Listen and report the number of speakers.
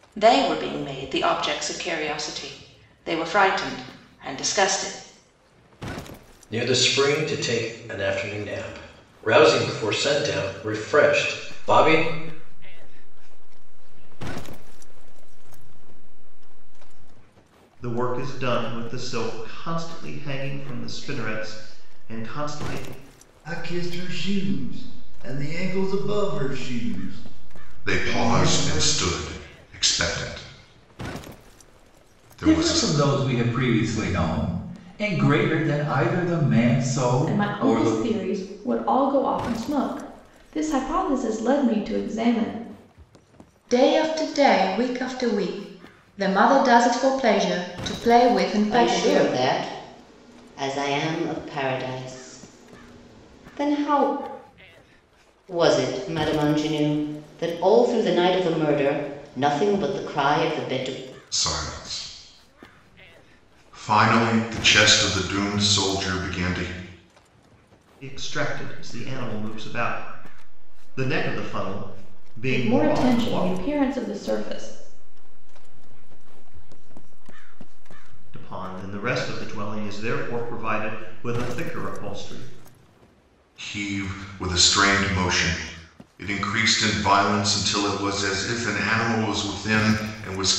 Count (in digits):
10